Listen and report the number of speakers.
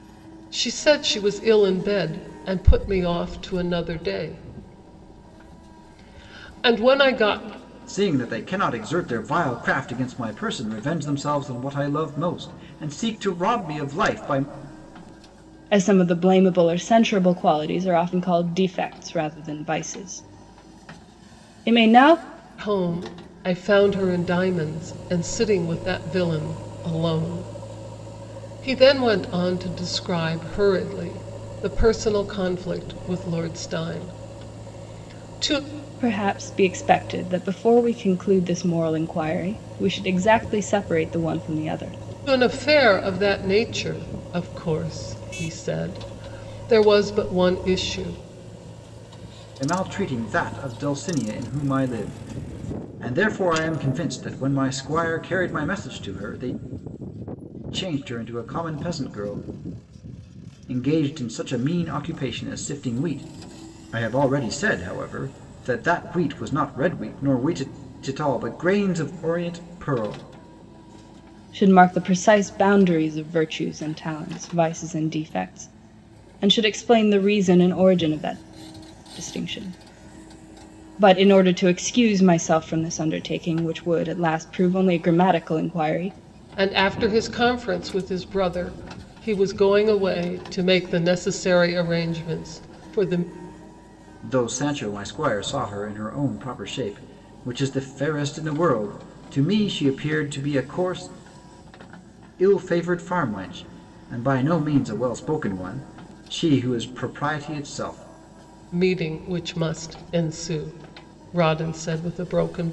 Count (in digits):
3